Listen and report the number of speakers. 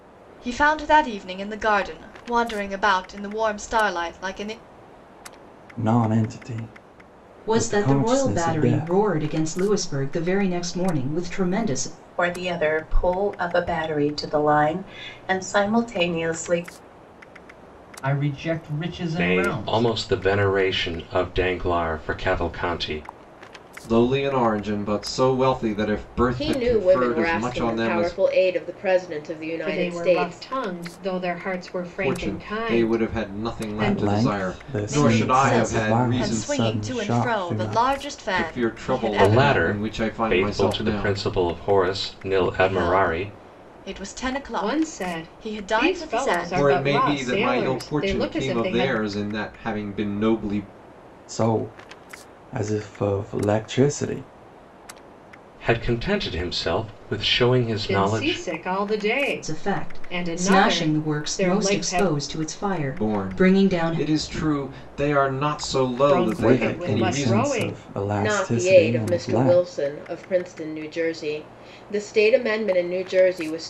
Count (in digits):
9